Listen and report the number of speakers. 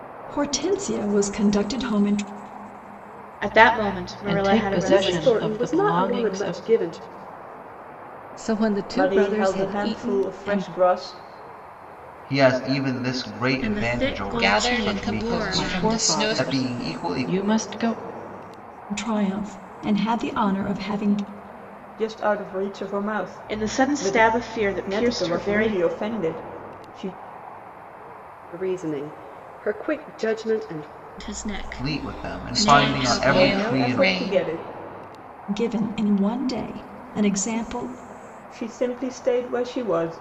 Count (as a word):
nine